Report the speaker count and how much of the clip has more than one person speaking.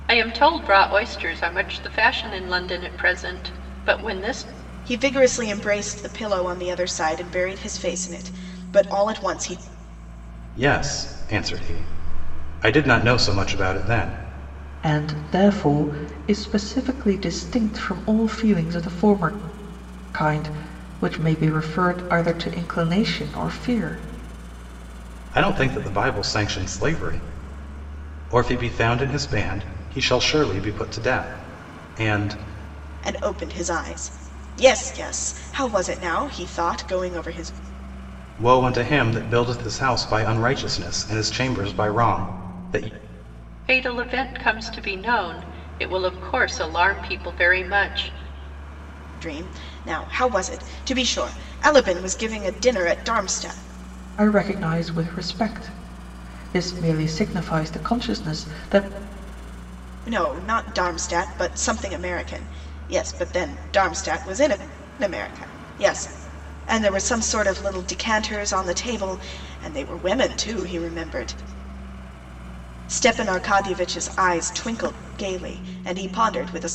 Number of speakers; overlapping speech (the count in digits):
4, no overlap